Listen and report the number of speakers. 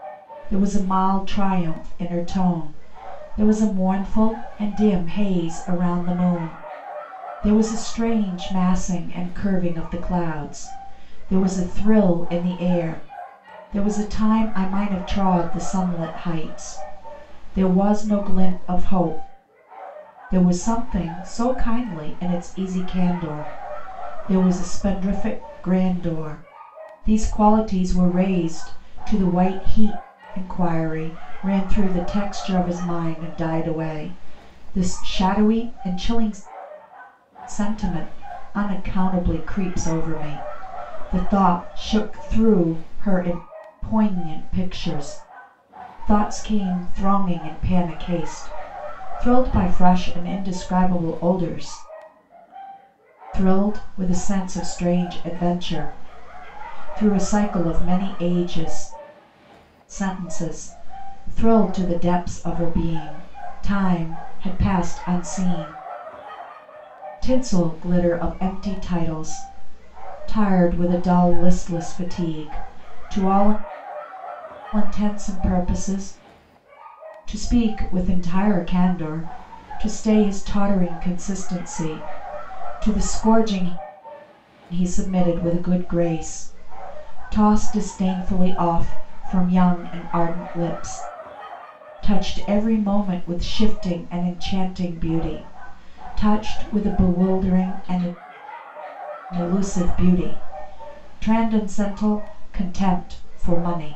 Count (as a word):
one